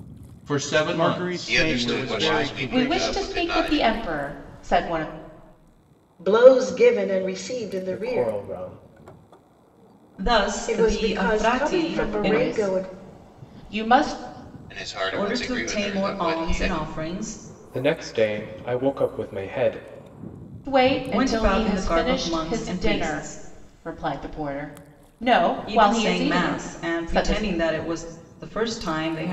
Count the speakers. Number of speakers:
seven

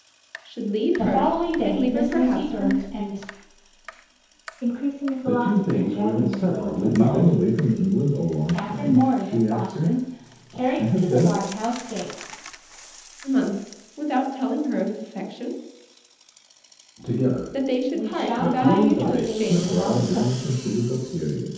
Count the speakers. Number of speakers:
five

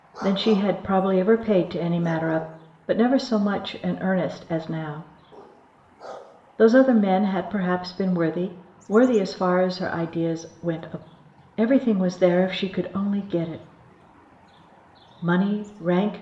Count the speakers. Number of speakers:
one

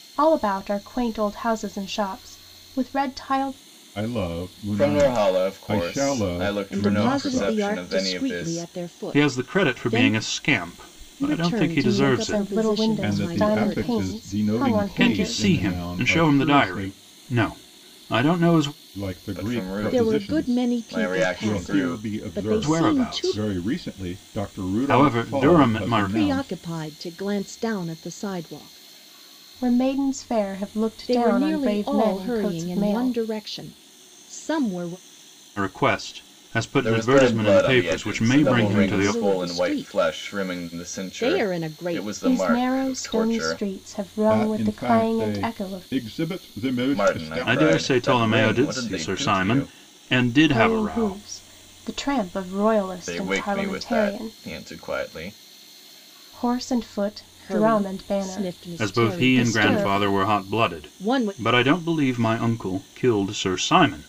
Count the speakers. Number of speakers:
five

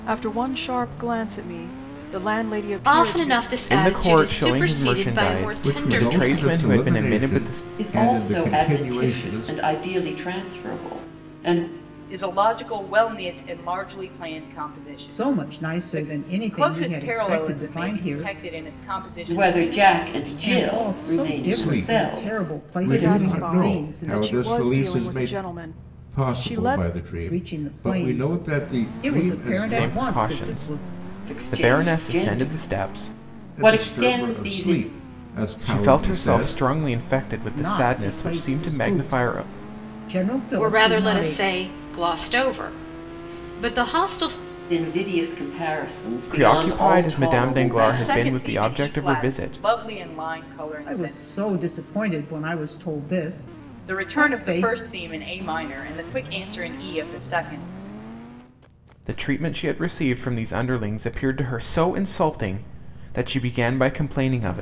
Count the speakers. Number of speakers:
seven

